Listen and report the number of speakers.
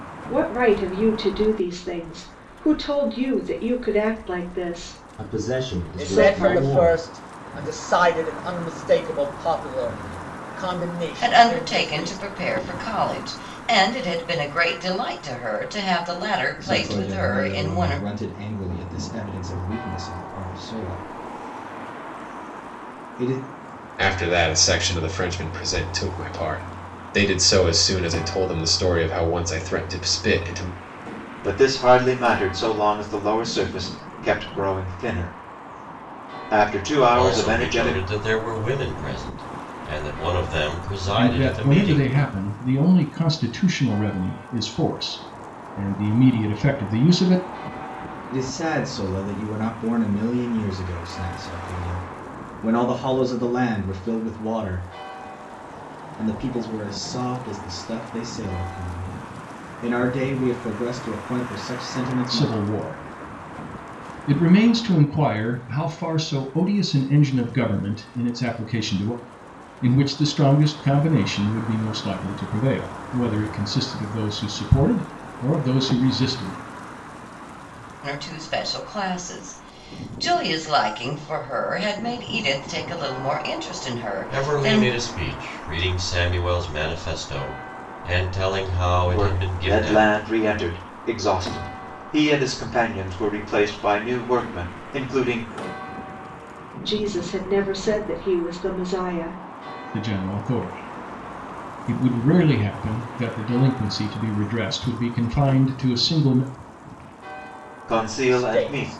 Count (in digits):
9